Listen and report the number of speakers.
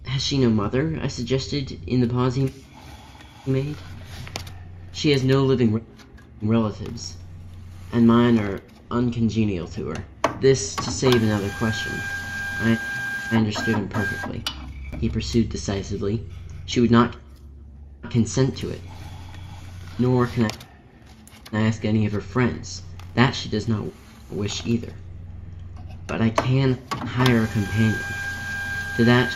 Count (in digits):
1